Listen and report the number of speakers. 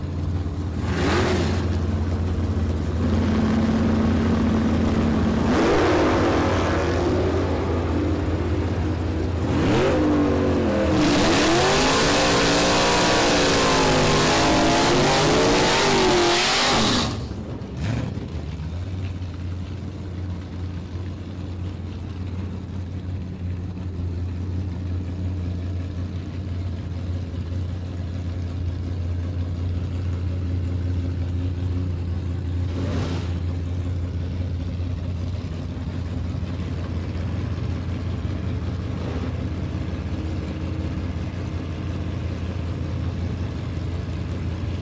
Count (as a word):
zero